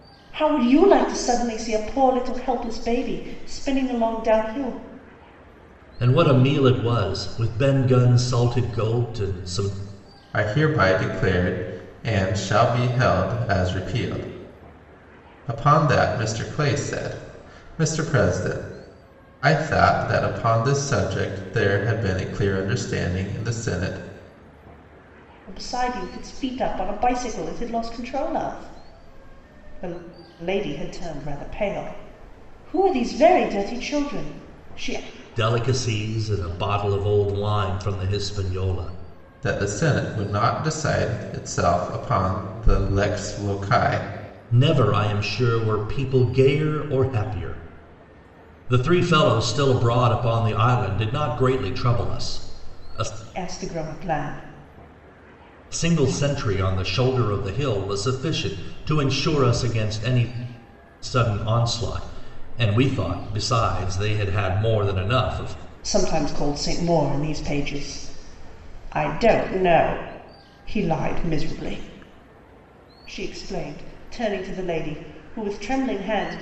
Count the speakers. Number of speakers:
3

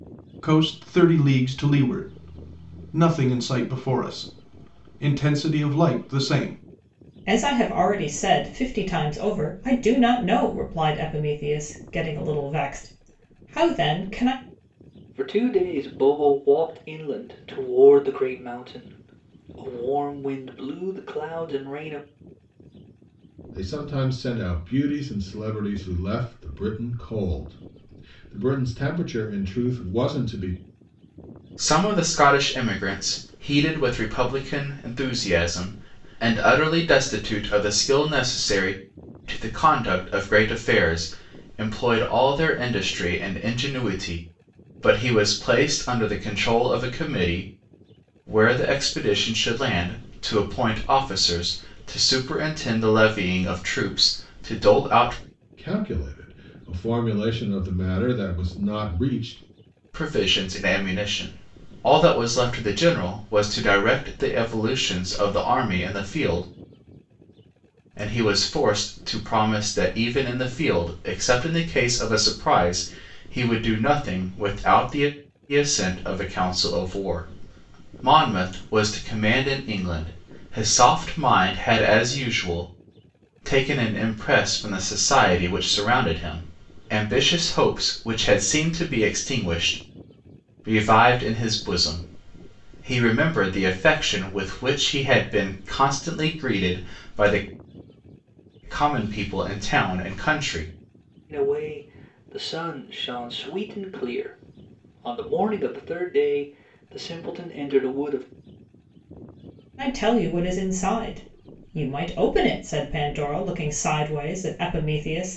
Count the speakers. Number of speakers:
5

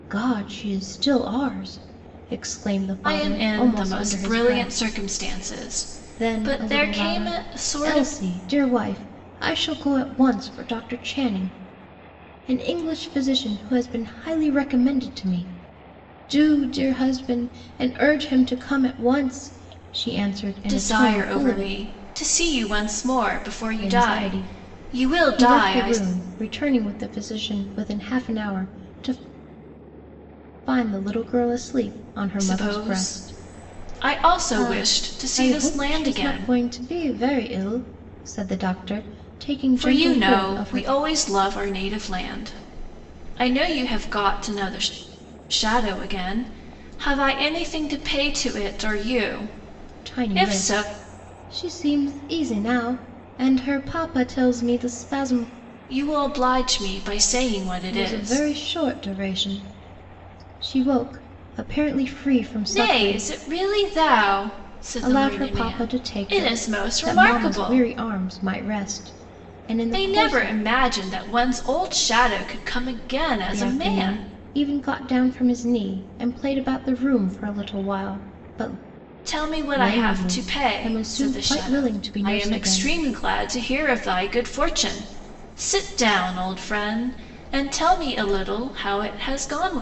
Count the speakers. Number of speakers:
2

